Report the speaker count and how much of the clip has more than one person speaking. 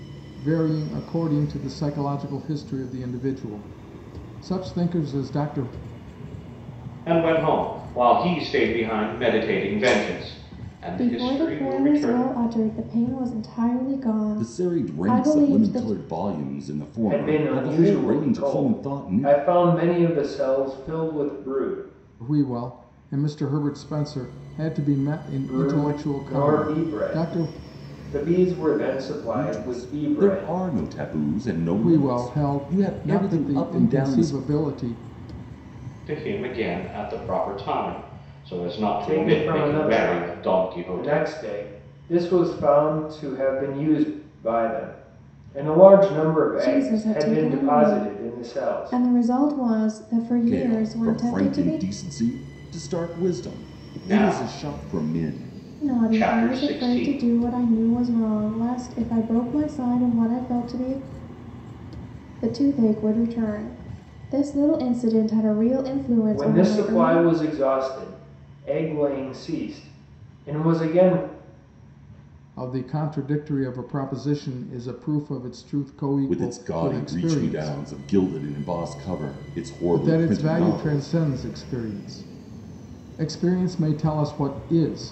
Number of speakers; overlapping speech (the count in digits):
5, about 28%